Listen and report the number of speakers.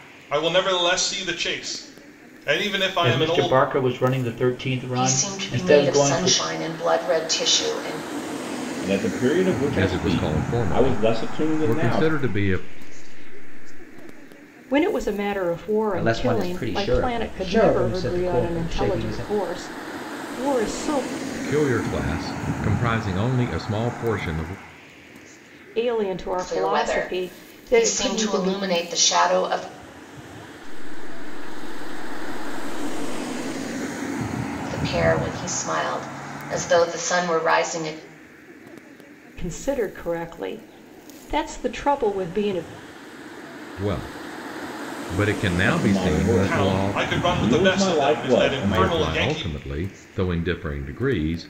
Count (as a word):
eight